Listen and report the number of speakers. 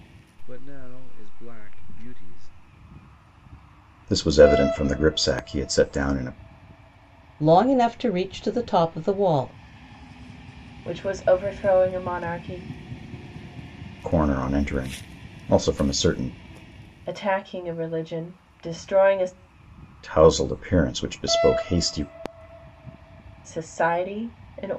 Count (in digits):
4